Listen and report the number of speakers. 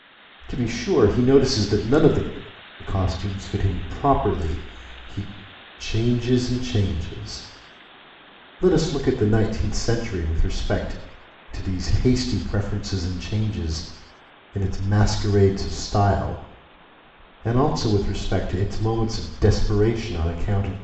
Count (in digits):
1